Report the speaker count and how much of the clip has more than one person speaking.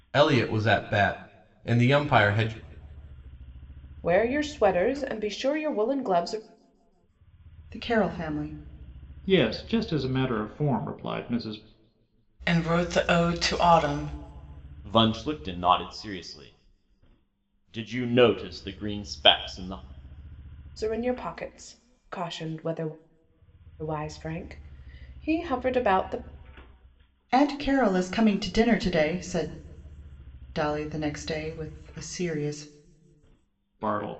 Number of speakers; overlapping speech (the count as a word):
six, no overlap